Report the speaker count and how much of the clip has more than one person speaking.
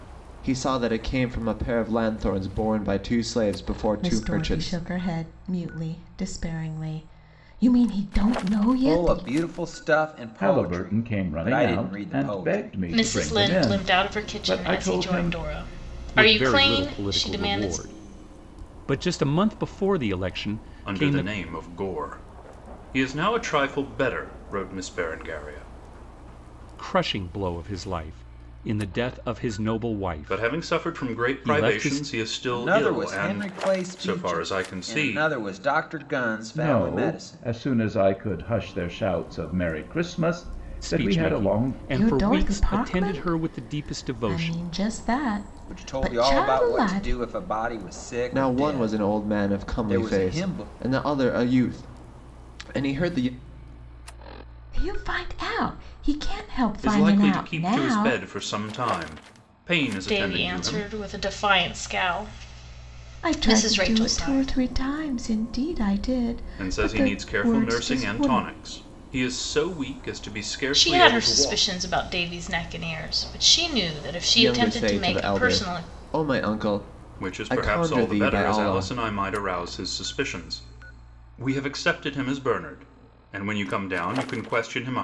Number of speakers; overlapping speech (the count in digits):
7, about 37%